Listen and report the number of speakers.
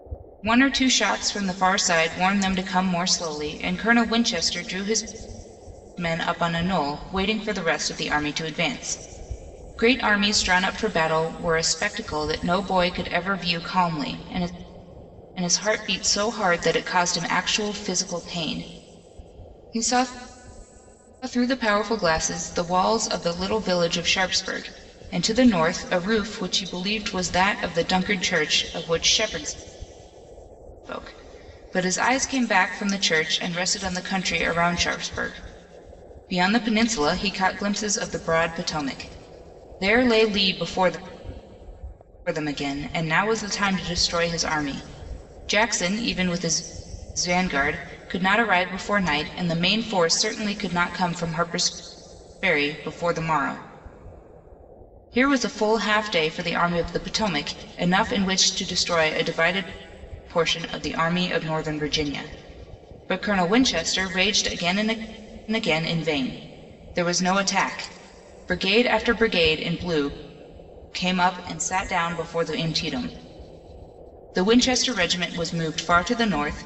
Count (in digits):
1